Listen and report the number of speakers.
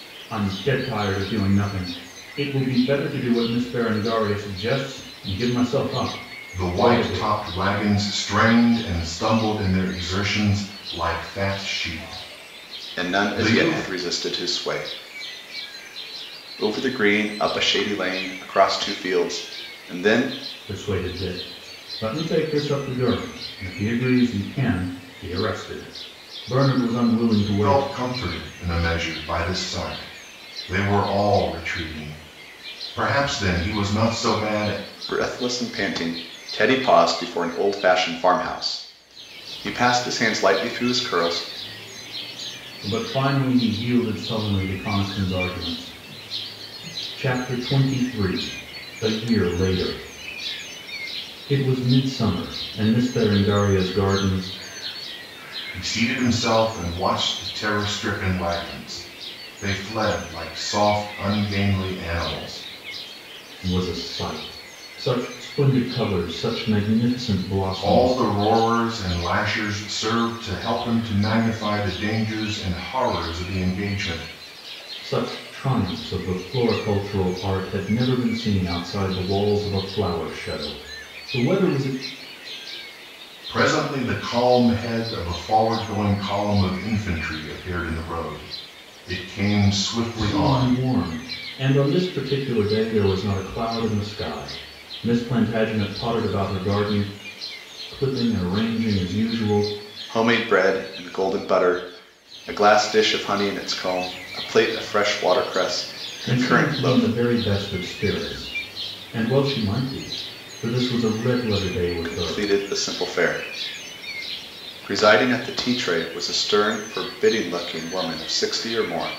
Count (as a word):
three